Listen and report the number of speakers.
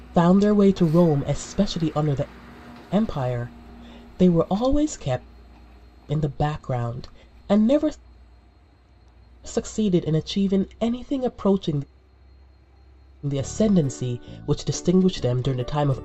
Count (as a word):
one